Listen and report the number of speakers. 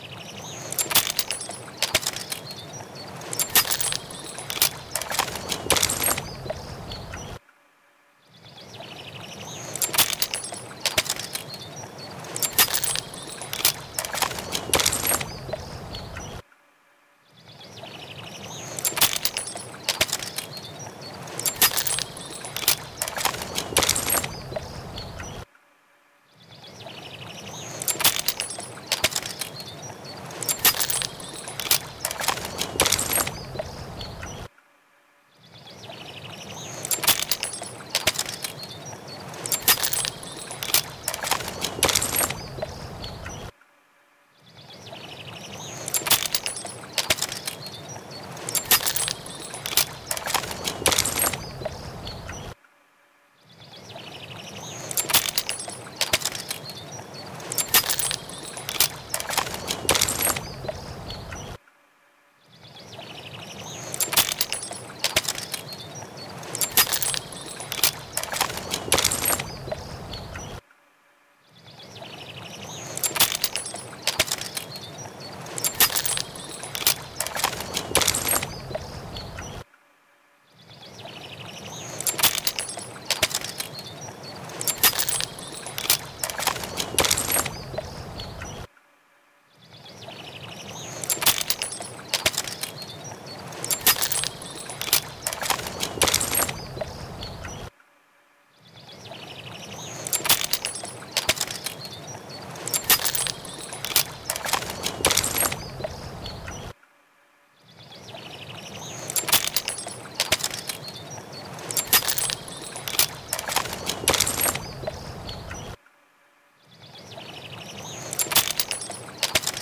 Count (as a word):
zero